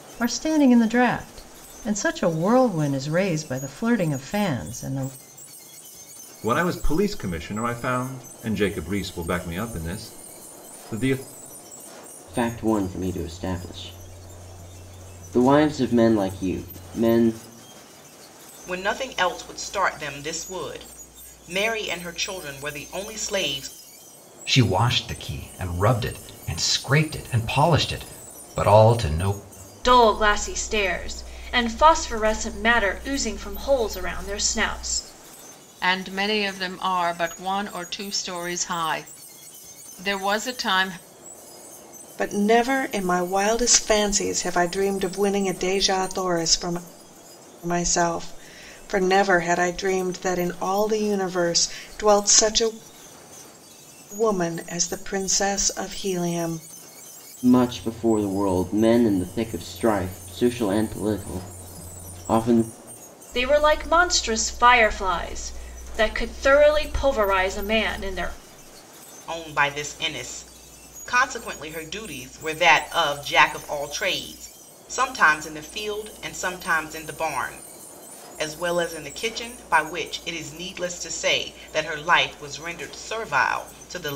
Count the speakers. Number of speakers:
8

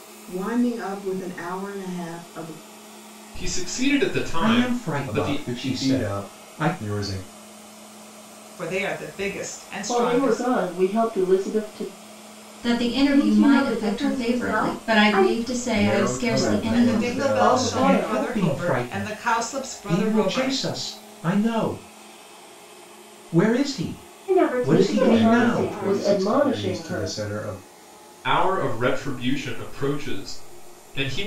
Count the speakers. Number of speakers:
8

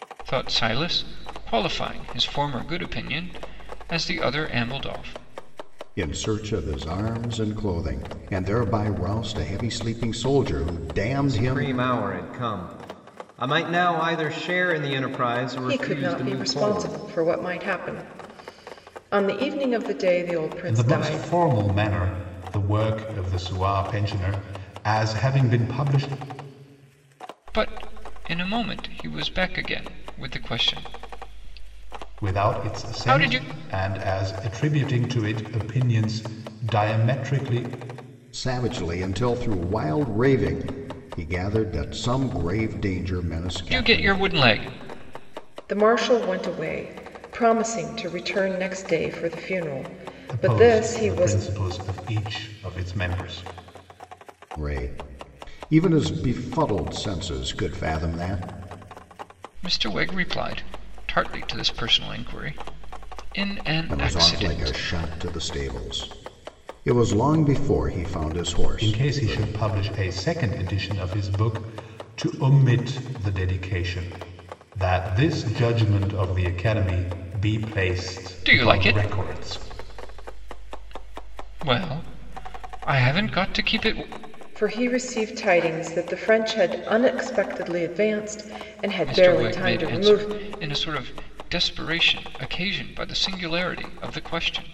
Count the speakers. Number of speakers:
5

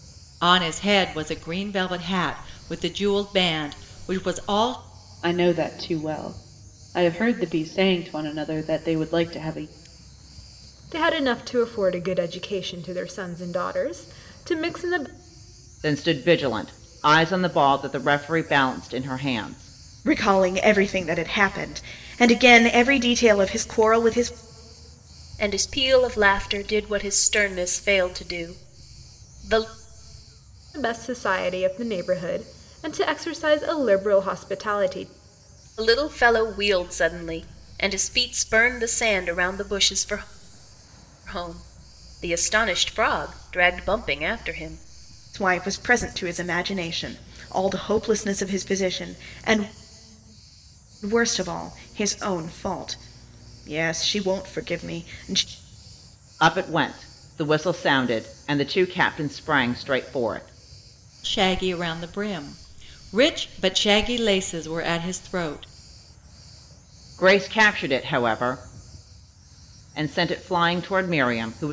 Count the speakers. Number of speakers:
6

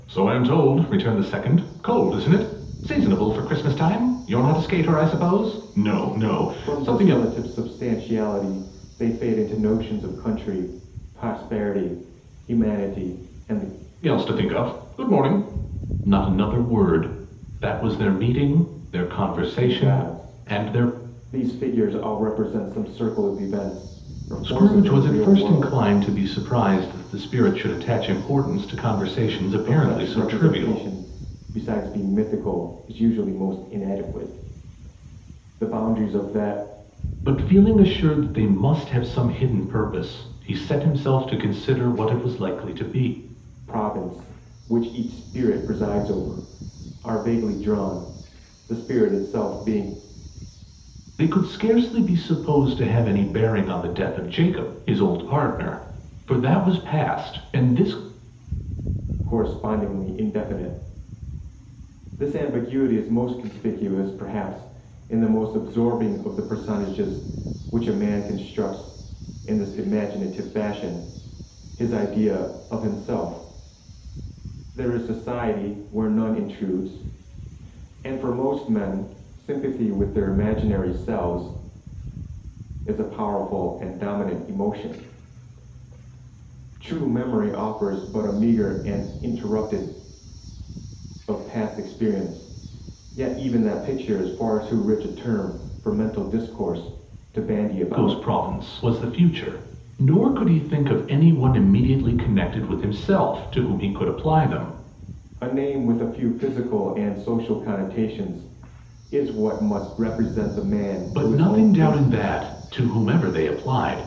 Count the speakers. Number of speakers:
2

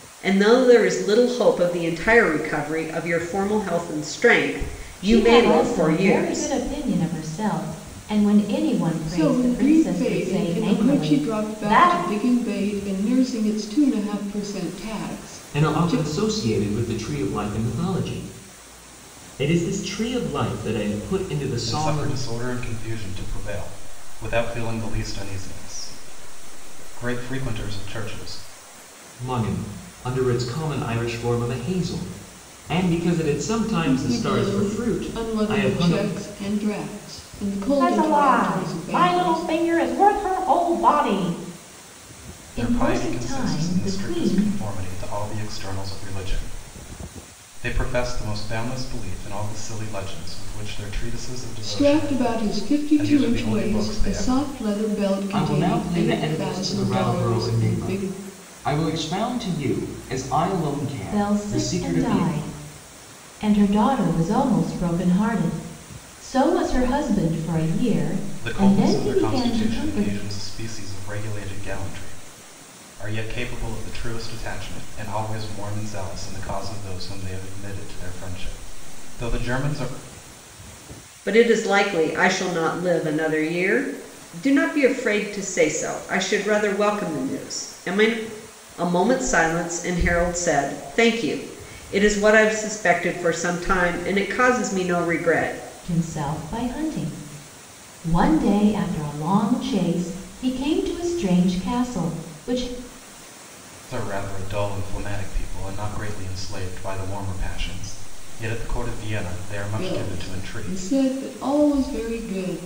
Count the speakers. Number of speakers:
5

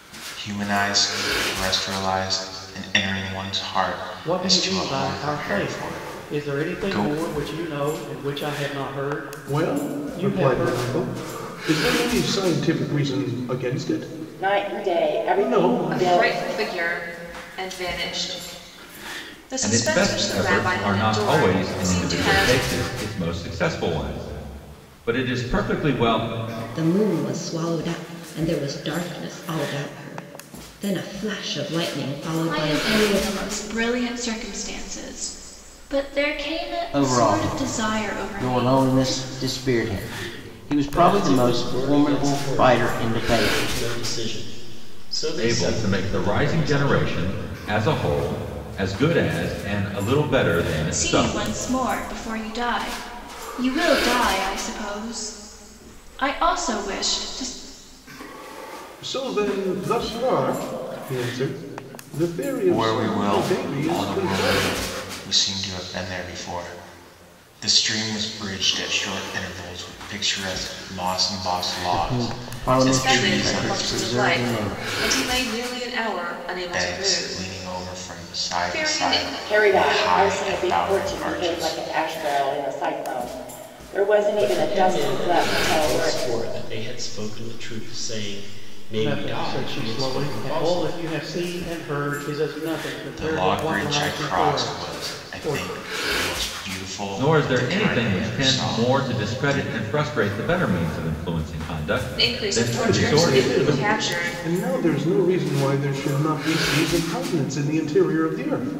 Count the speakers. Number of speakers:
10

